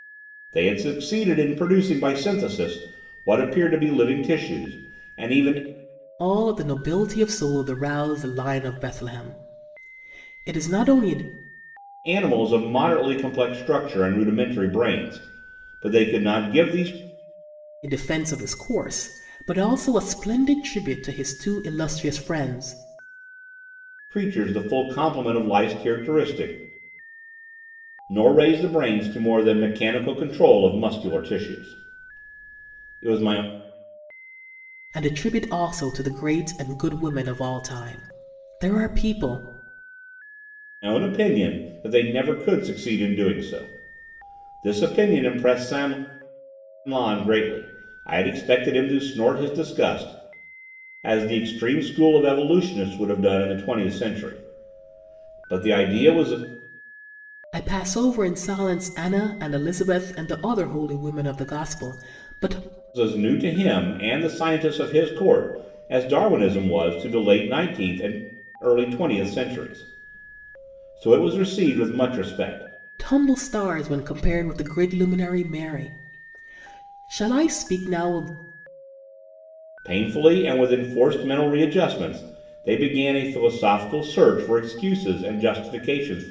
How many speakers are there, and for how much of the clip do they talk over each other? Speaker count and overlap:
two, no overlap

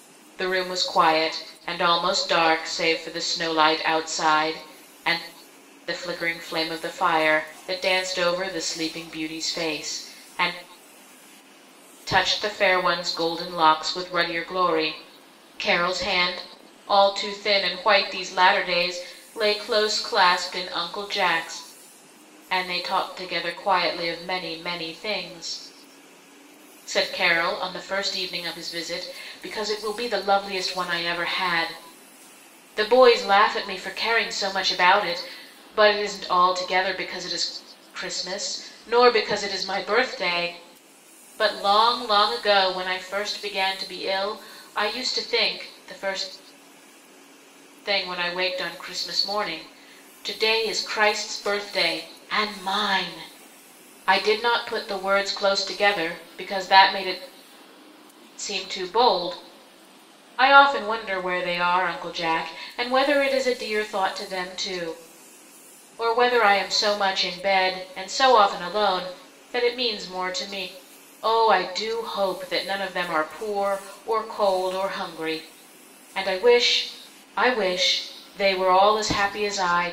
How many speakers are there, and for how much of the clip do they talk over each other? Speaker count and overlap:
one, no overlap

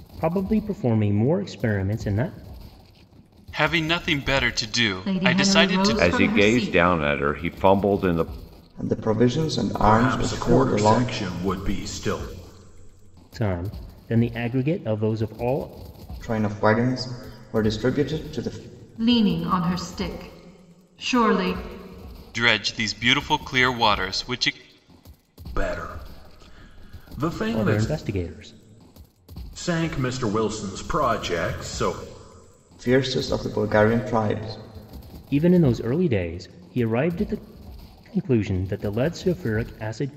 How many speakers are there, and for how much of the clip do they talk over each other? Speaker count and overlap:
six, about 9%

